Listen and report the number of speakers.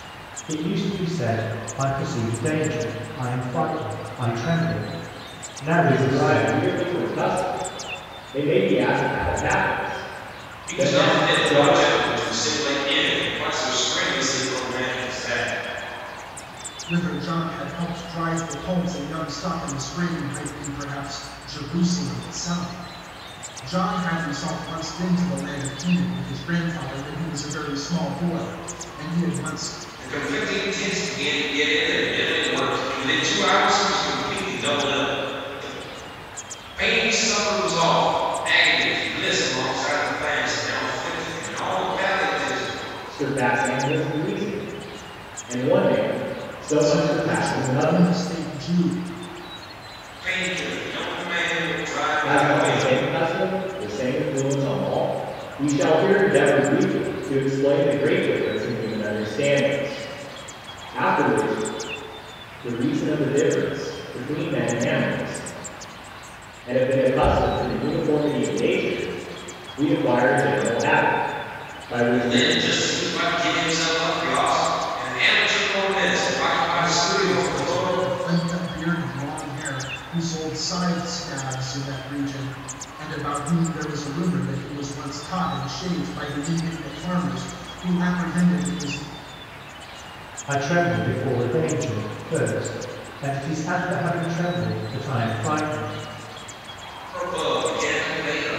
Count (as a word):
four